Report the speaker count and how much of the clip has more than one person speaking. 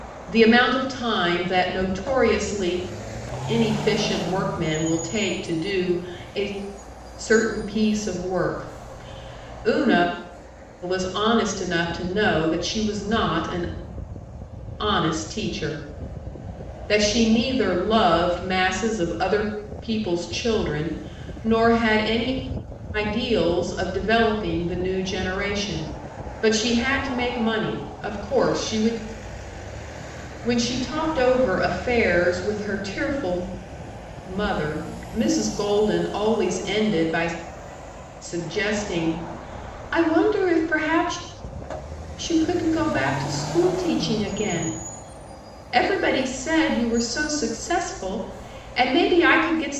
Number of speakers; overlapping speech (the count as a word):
one, no overlap